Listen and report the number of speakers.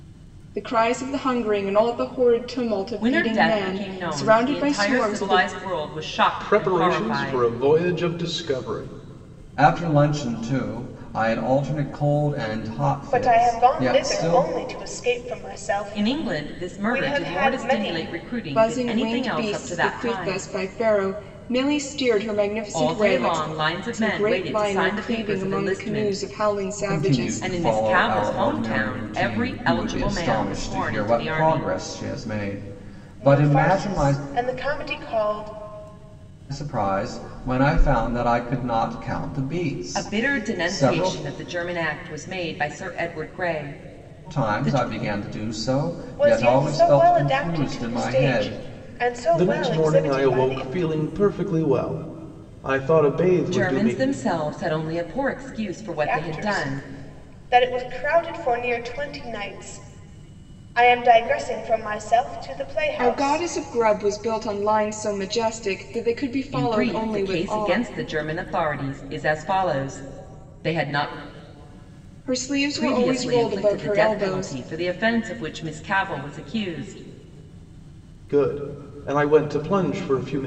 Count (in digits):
5